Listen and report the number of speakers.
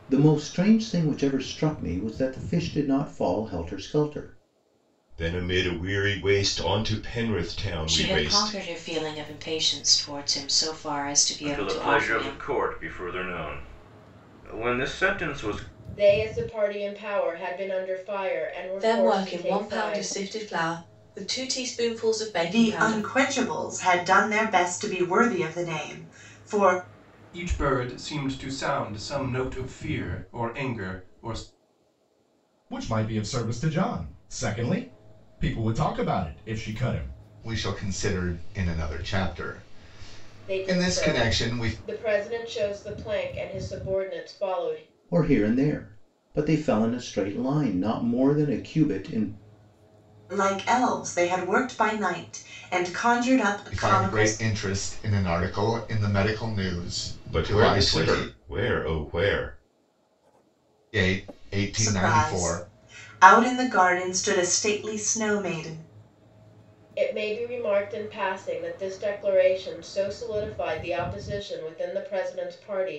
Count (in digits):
10